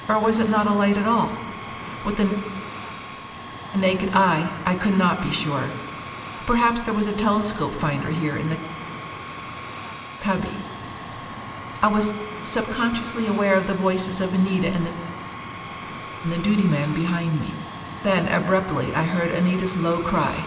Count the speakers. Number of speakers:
1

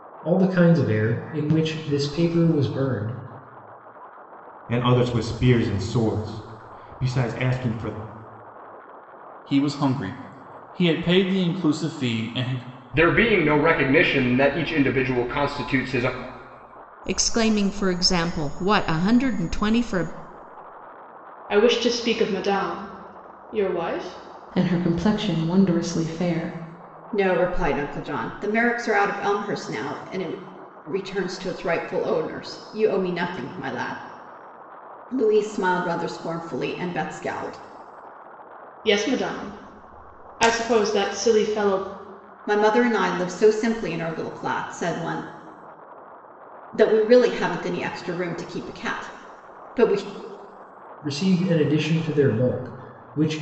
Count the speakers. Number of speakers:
8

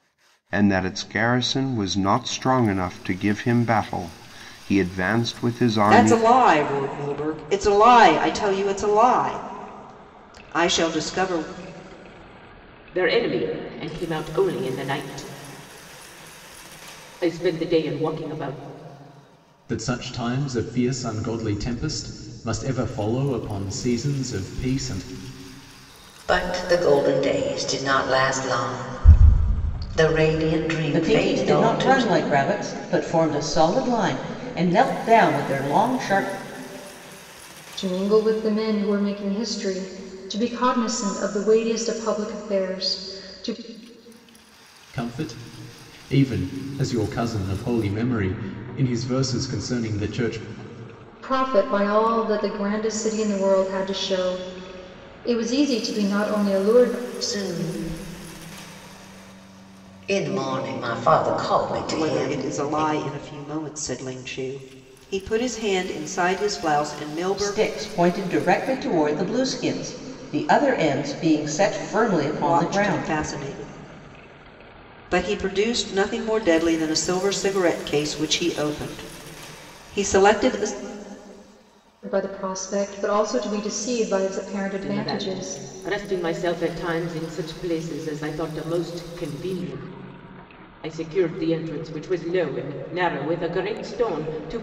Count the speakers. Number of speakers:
7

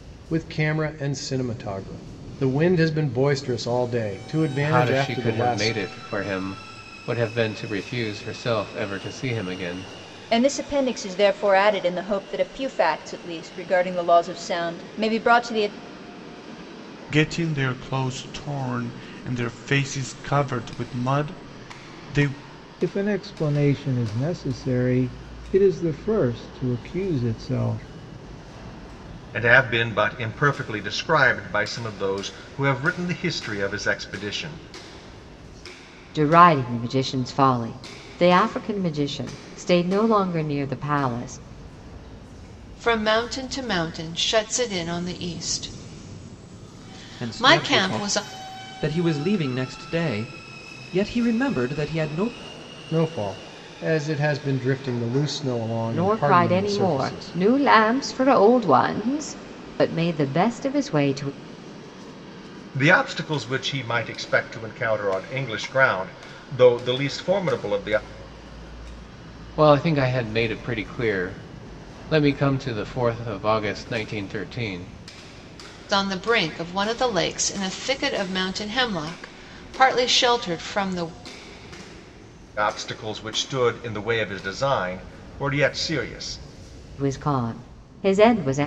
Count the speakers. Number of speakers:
9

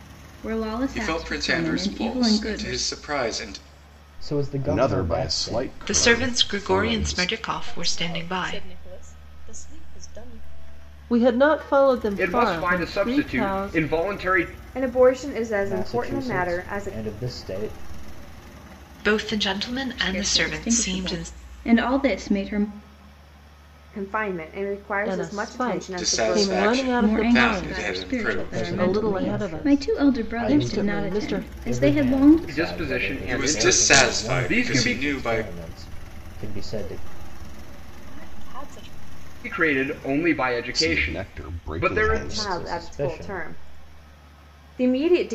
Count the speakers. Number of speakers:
9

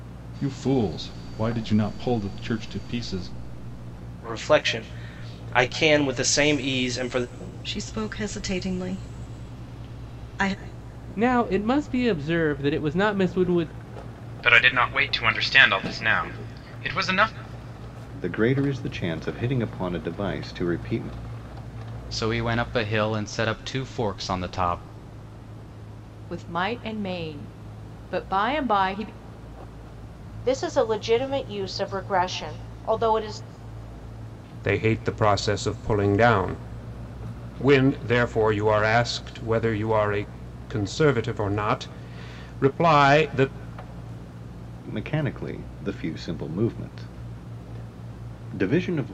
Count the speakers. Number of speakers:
10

